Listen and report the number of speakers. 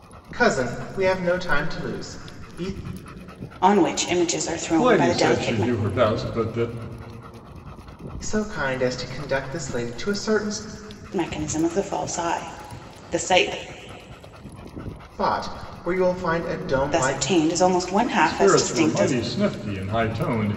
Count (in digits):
3